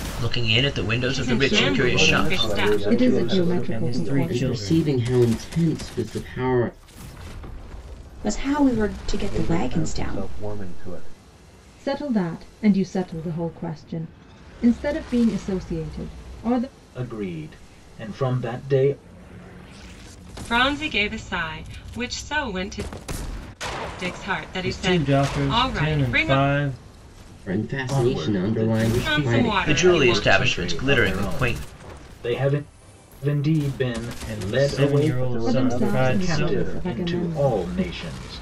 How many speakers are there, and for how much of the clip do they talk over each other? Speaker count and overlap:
8, about 37%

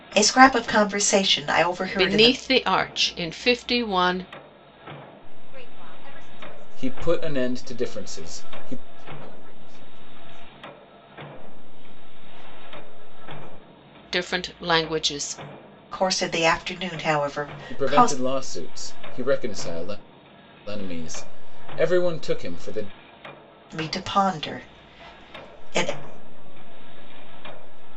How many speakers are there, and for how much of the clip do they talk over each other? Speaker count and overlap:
4, about 9%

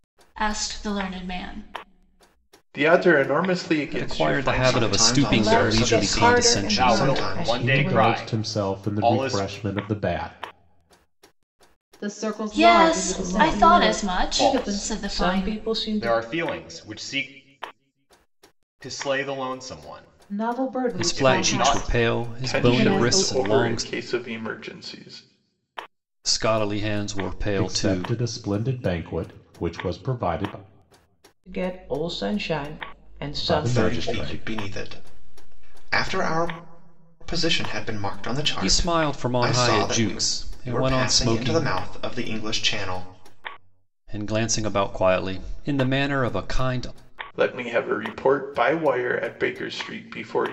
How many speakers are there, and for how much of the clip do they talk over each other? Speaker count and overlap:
8, about 34%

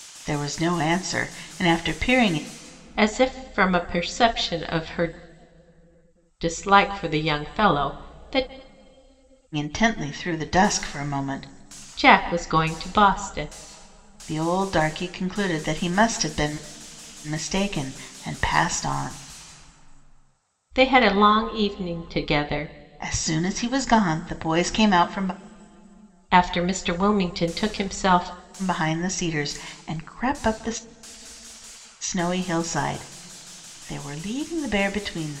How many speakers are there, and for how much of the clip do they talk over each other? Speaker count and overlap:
2, no overlap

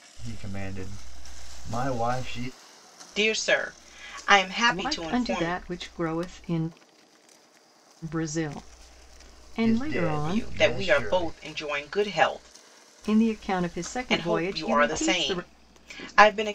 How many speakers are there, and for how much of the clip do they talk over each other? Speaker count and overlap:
3, about 24%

